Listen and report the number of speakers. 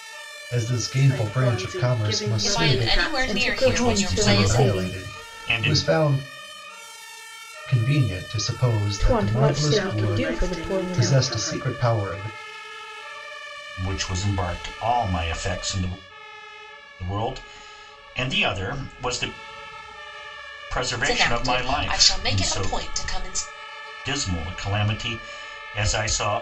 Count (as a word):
five